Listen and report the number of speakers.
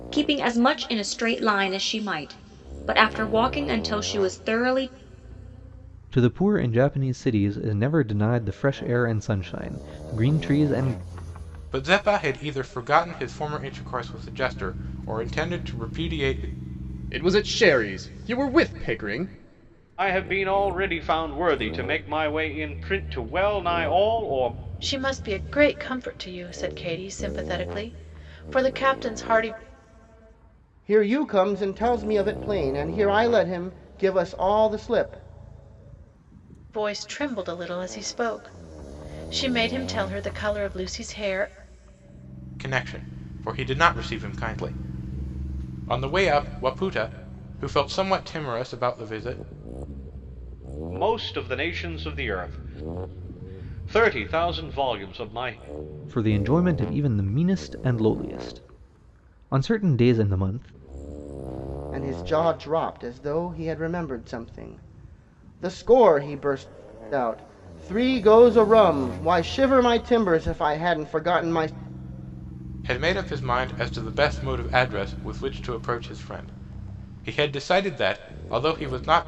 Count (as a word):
seven